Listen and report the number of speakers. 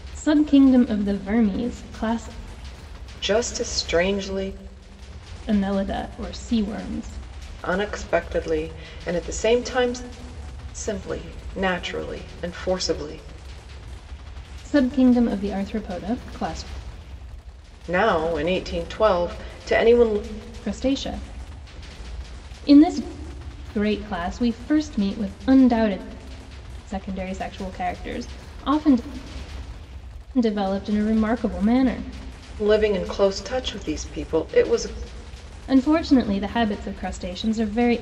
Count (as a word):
two